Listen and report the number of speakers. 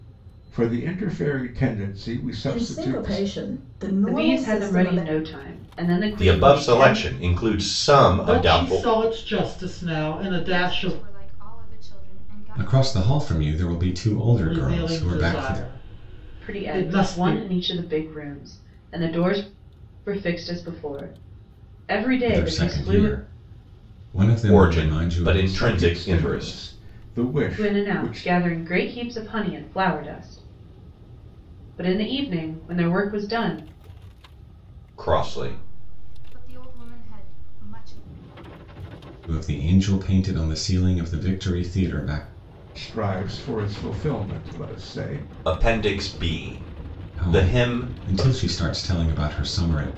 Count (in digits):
7